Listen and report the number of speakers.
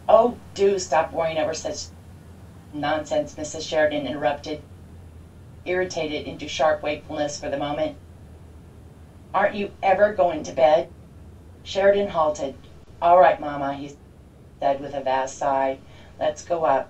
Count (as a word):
one